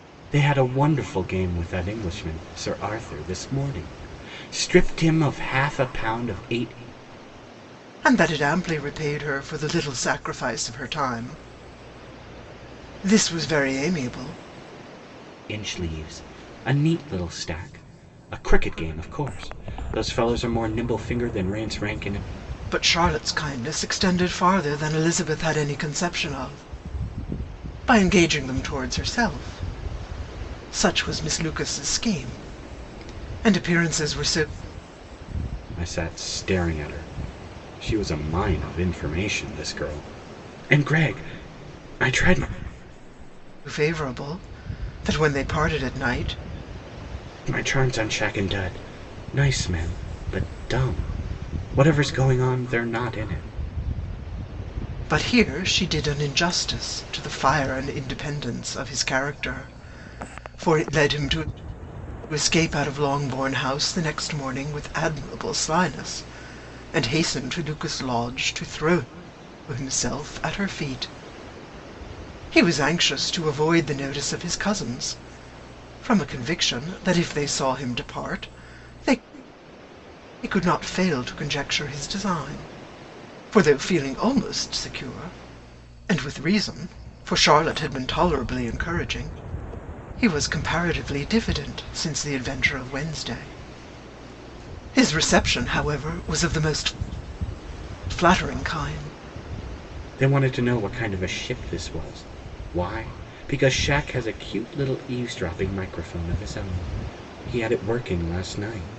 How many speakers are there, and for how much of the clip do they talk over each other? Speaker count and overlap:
2, no overlap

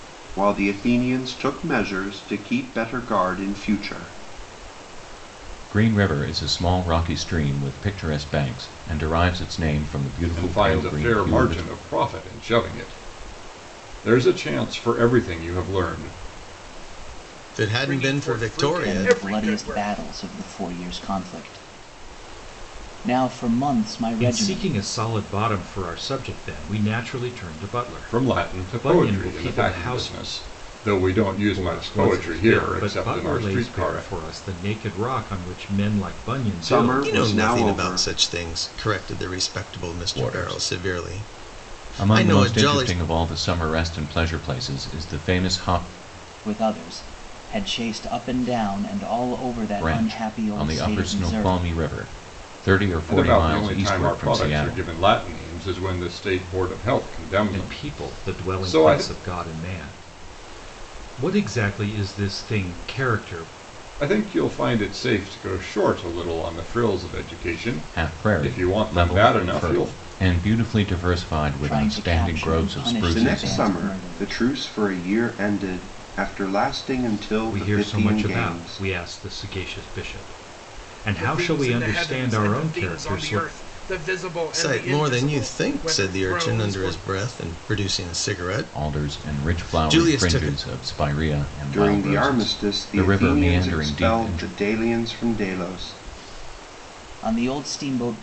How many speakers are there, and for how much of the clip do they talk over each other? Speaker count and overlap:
7, about 35%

